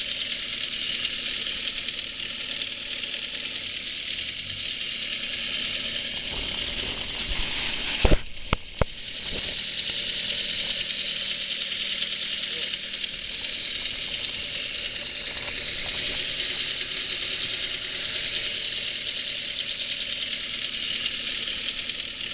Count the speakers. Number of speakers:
zero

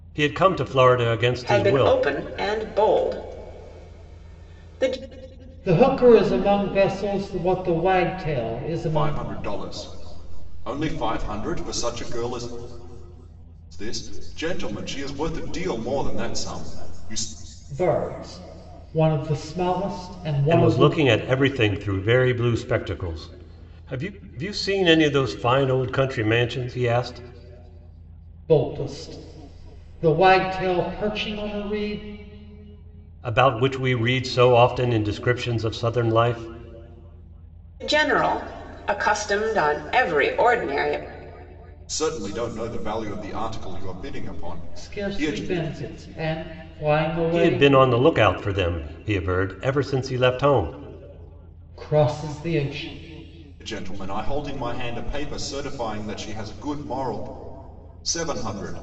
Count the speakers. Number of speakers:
four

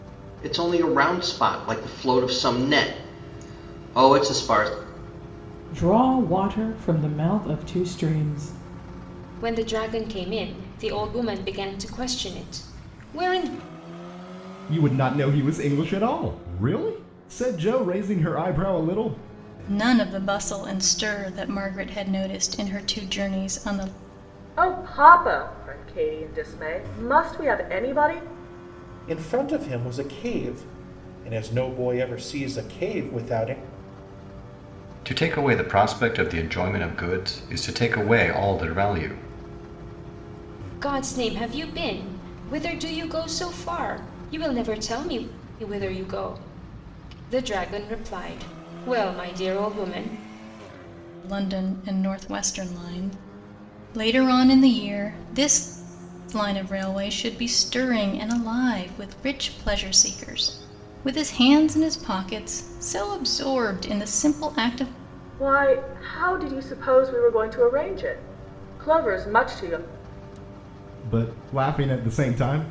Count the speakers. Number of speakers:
eight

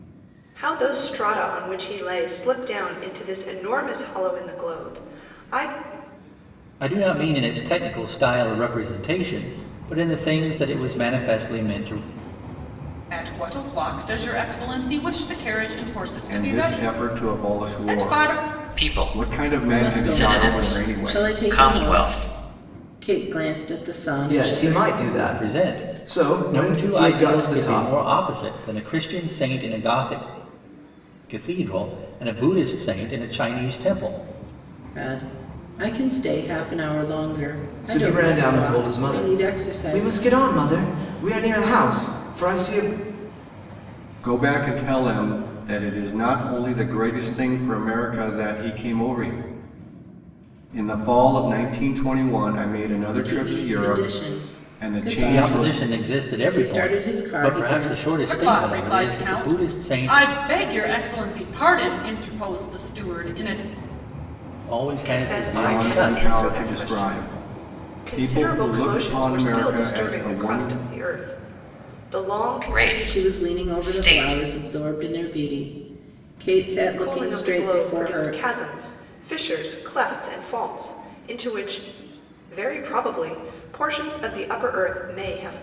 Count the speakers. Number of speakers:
seven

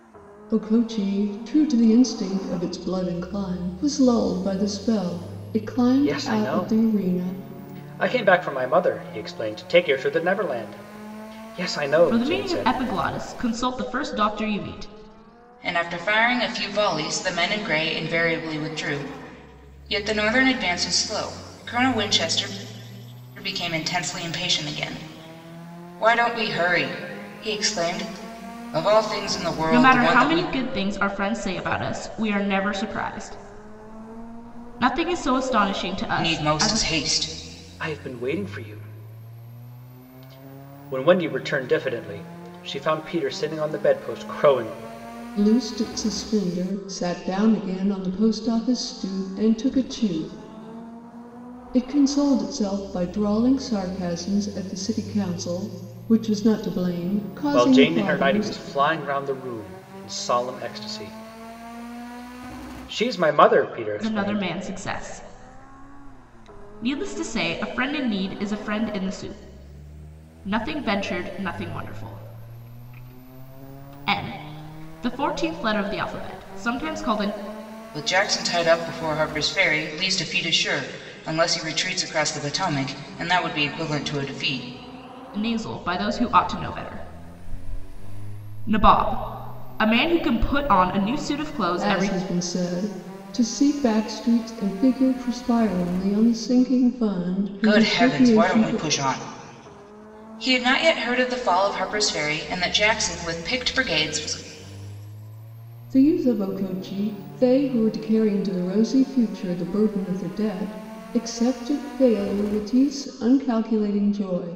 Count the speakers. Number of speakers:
four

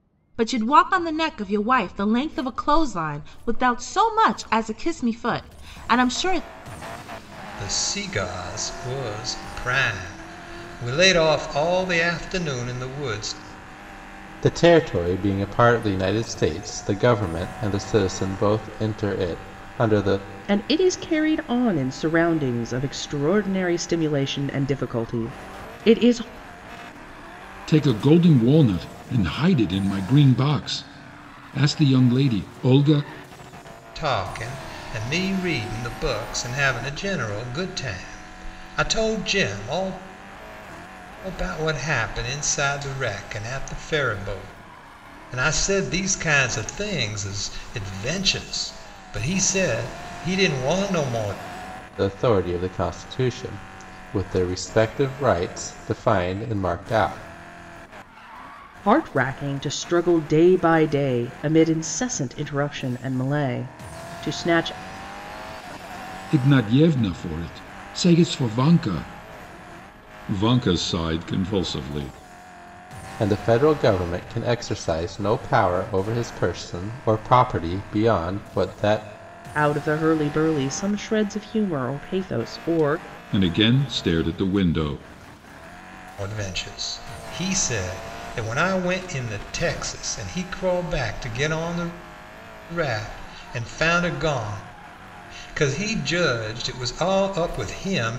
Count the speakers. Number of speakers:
five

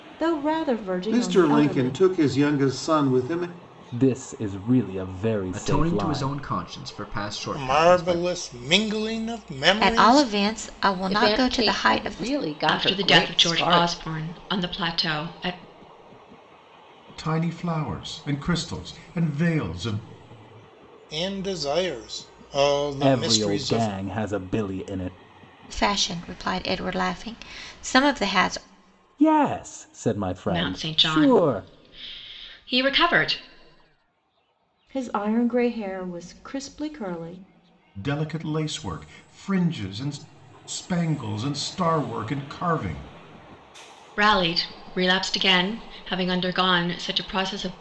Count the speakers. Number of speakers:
nine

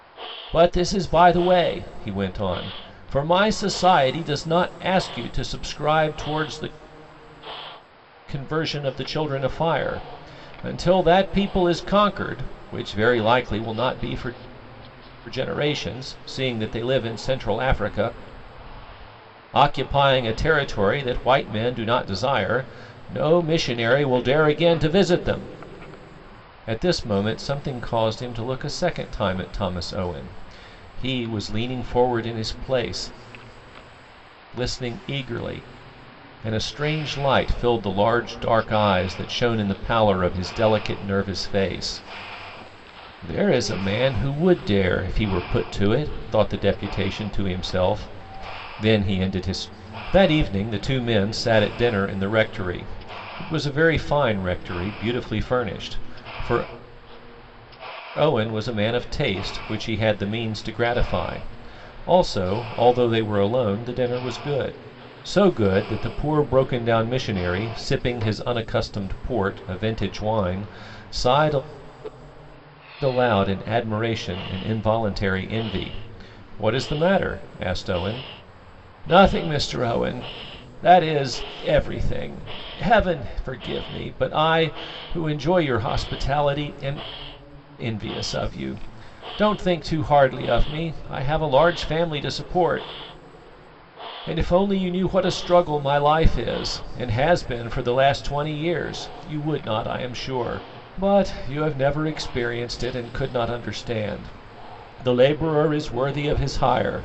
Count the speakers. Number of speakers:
one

